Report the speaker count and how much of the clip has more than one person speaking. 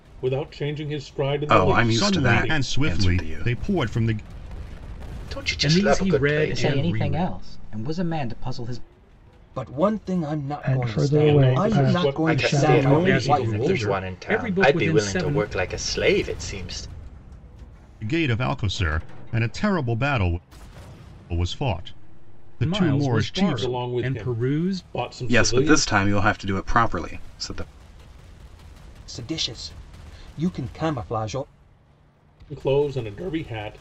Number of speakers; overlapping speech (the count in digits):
8, about 35%